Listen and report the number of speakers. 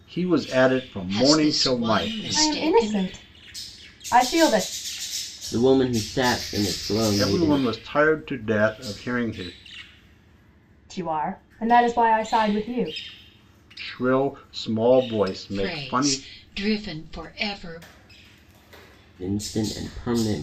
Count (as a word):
four